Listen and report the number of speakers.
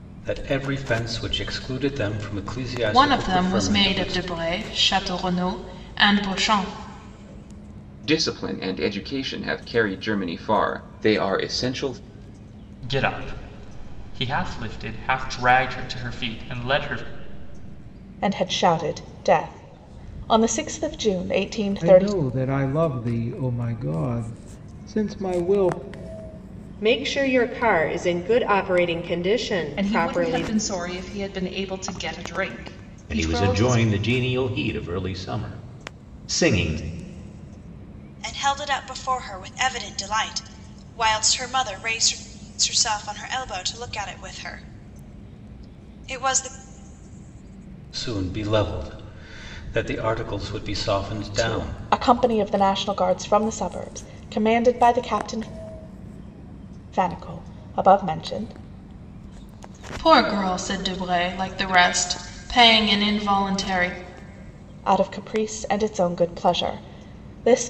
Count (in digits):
10